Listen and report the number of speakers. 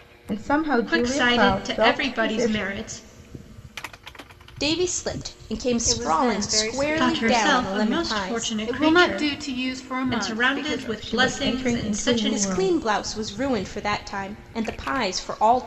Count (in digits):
4